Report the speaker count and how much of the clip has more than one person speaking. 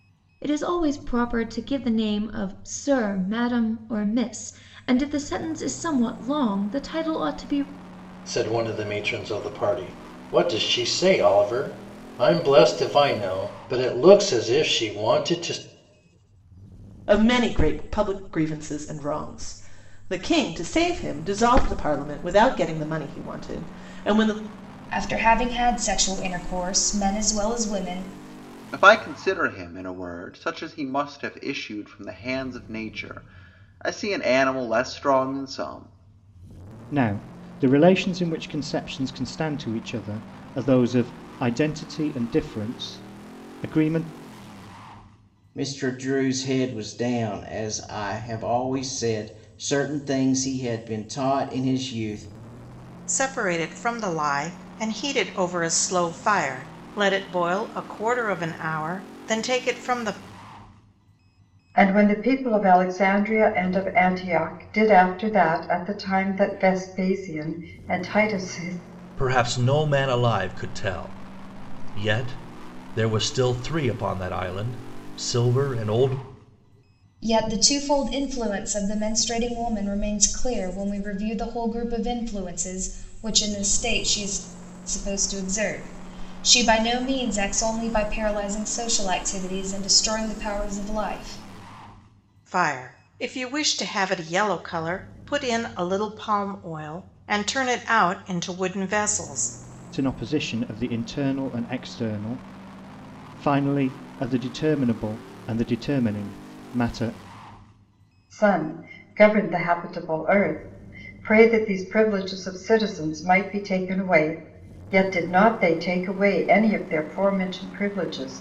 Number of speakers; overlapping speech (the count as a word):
ten, no overlap